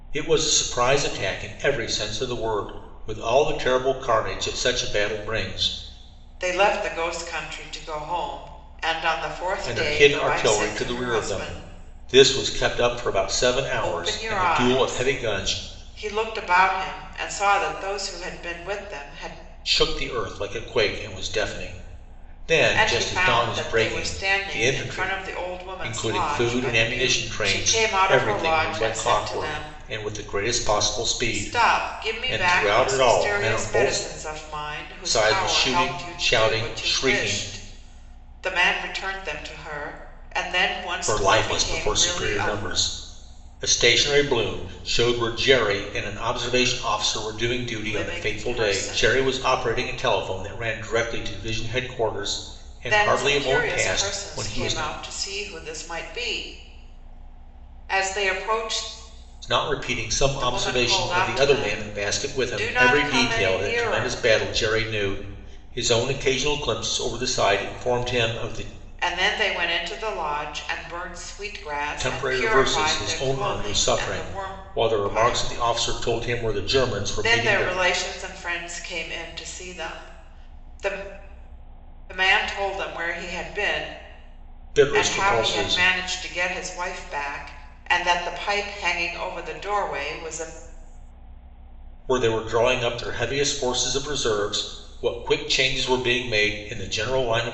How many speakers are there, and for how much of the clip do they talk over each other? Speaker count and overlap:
2, about 31%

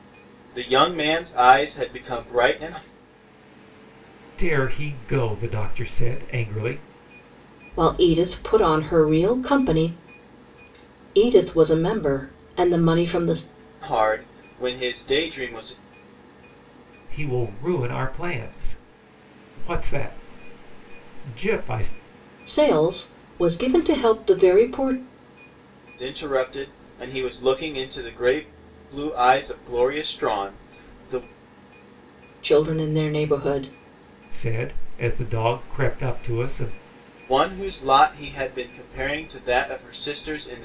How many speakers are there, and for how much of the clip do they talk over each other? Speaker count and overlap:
3, no overlap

